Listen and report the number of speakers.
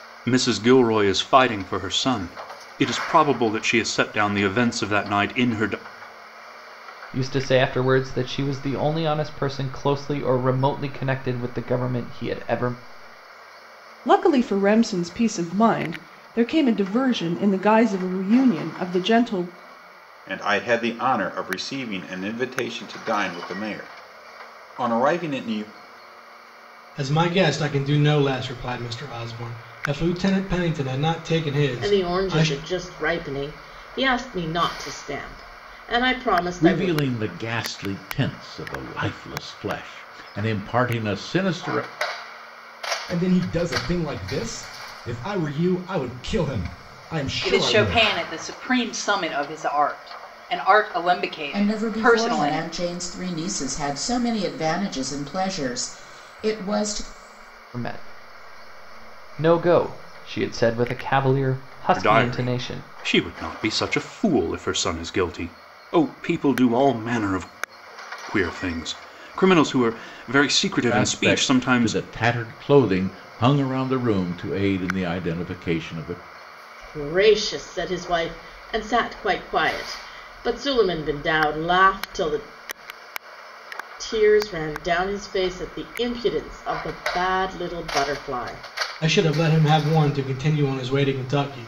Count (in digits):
10